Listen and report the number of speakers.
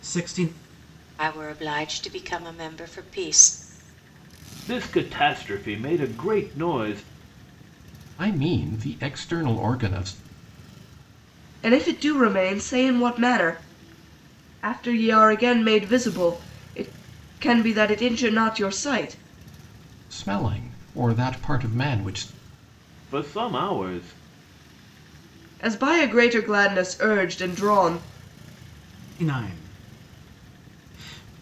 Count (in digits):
5